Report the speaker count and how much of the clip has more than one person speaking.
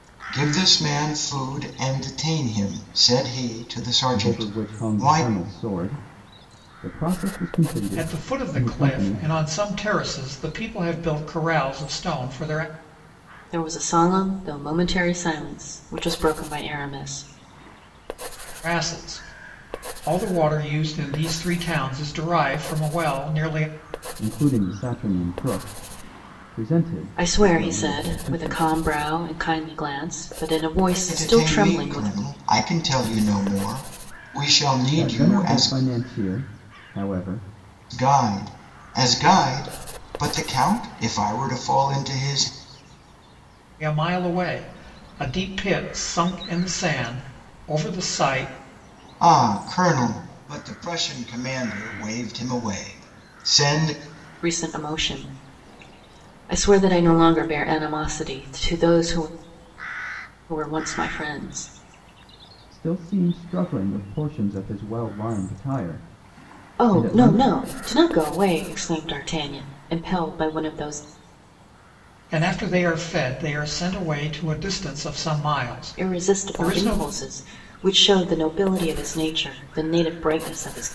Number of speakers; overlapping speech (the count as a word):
four, about 9%